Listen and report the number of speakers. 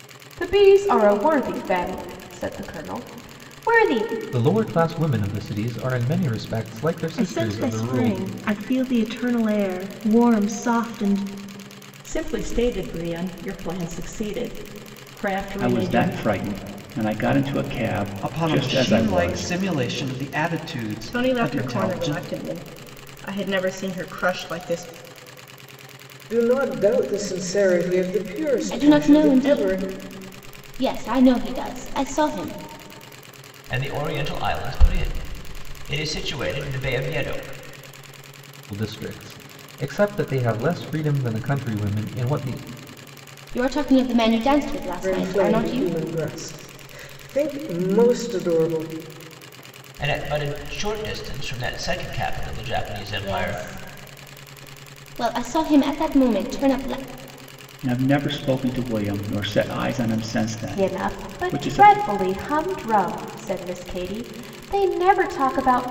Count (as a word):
ten